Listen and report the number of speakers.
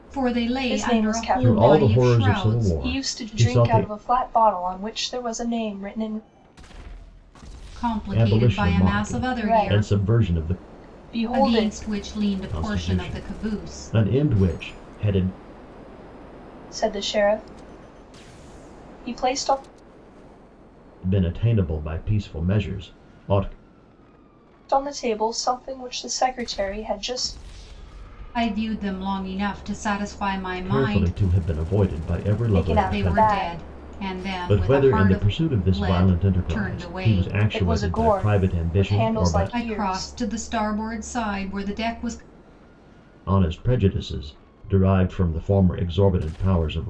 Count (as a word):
three